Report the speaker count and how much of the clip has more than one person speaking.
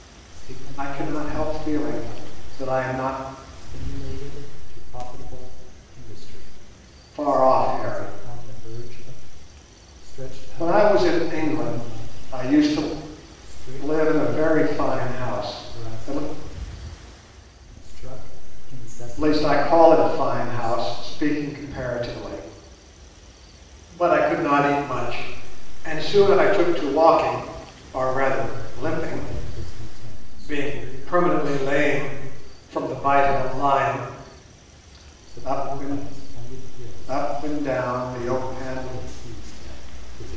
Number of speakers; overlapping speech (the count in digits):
2, about 43%